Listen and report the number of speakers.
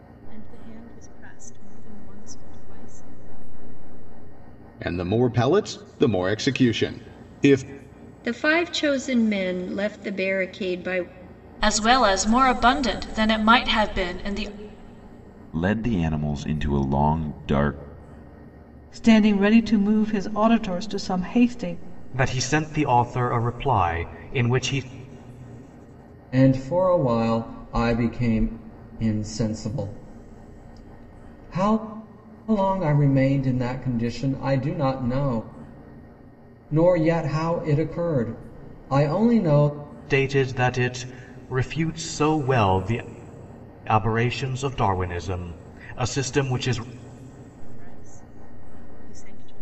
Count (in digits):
8